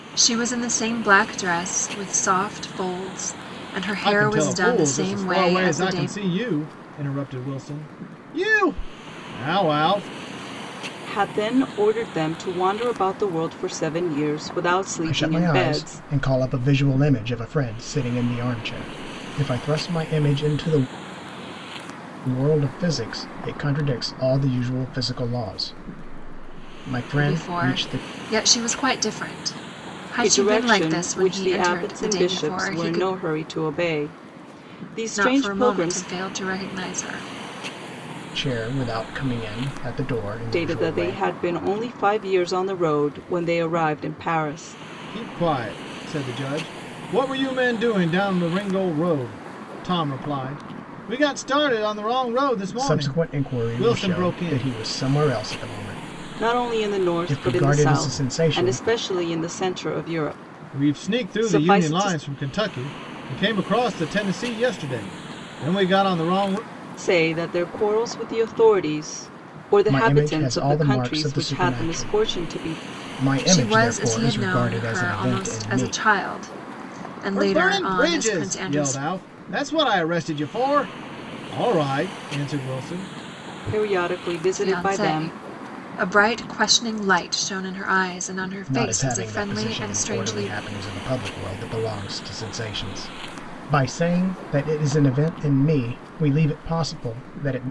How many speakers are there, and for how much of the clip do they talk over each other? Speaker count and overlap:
4, about 25%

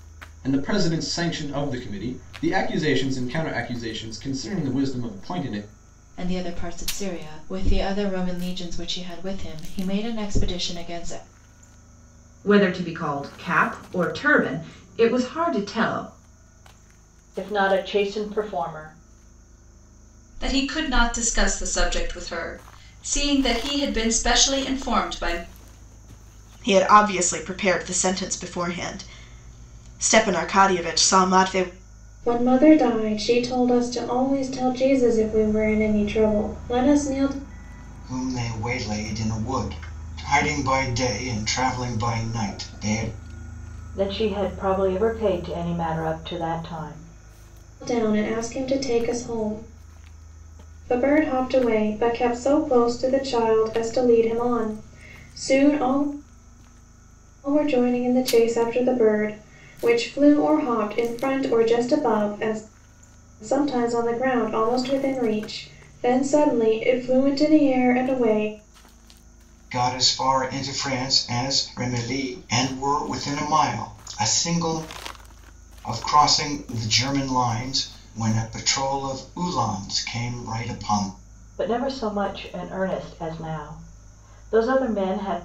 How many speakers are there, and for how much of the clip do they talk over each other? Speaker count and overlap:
8, no overlap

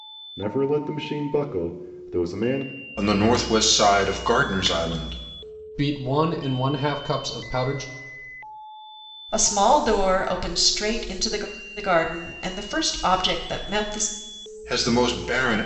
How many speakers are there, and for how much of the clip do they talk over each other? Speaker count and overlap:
4, no overlap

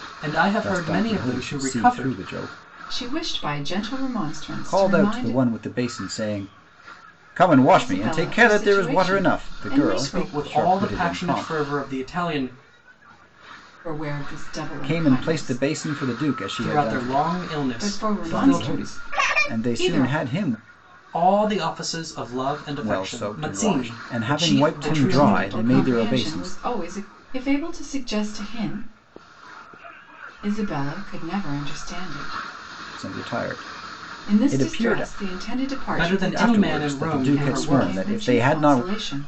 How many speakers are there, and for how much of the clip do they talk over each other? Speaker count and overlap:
3, about 45%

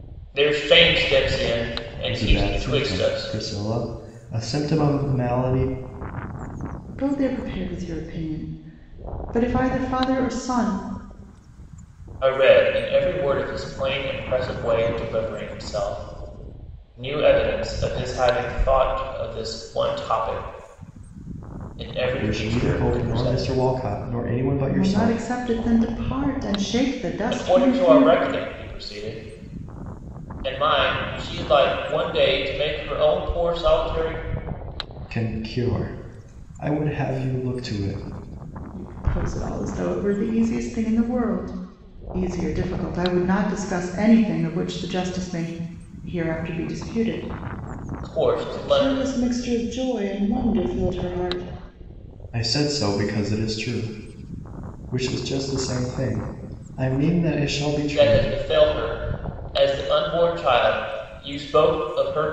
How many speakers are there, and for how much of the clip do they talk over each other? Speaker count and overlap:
3, about 9%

